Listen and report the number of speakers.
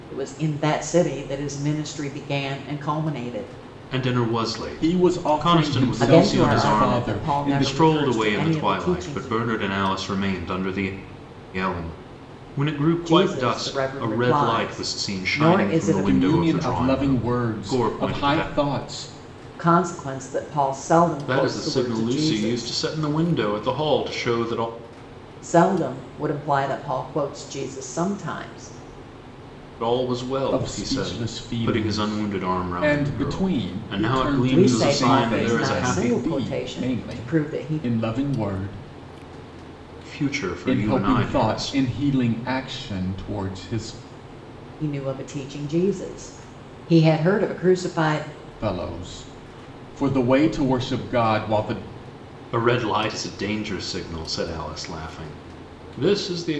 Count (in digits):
3